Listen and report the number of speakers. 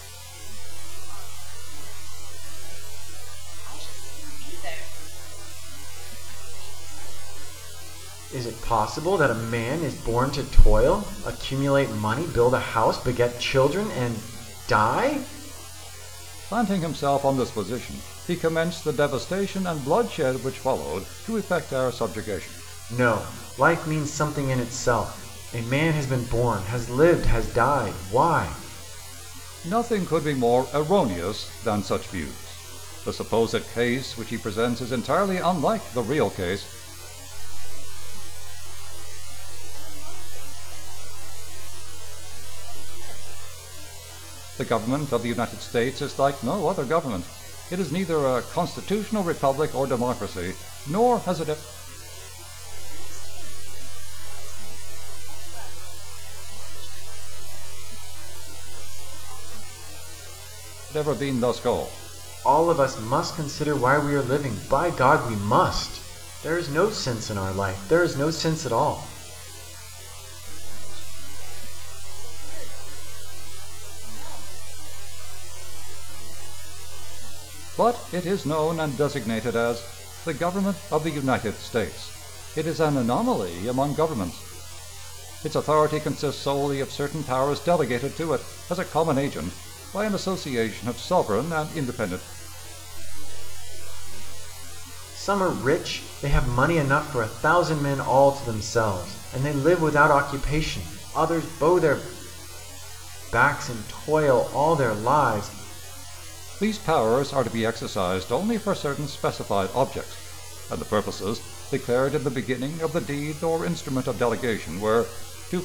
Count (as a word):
three